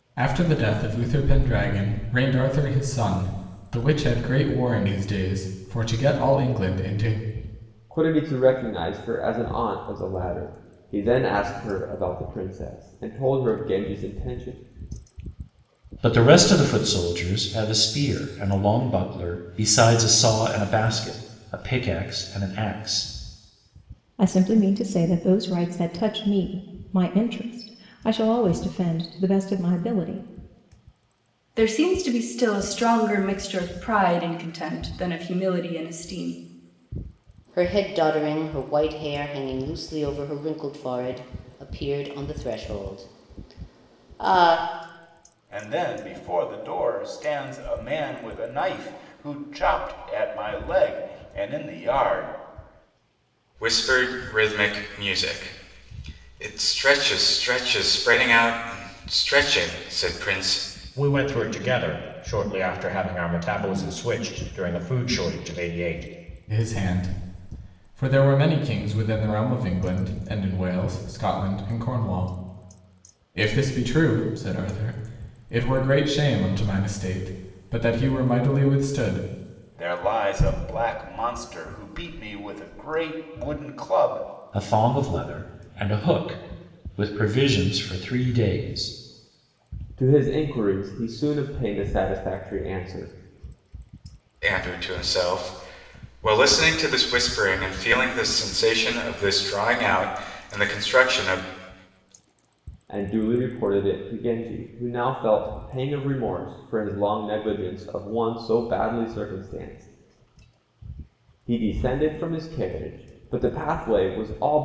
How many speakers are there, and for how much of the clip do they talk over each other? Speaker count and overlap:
nine, no overlap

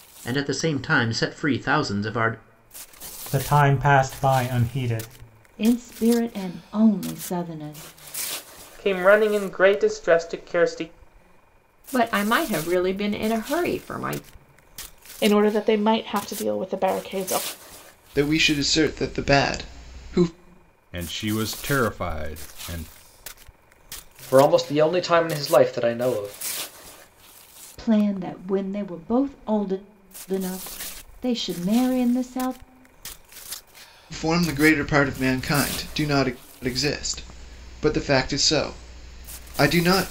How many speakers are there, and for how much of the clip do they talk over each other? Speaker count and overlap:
nine, no overlap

